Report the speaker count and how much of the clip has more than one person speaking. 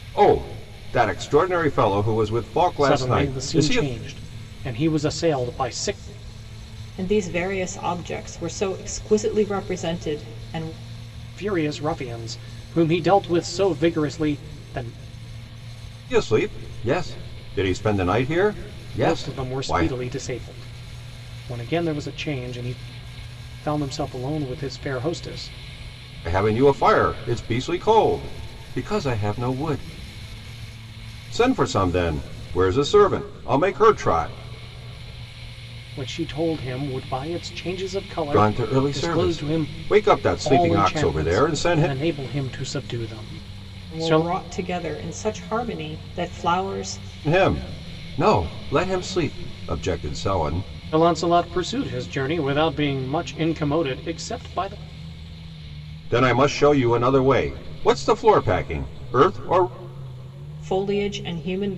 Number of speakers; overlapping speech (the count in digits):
3, about 9%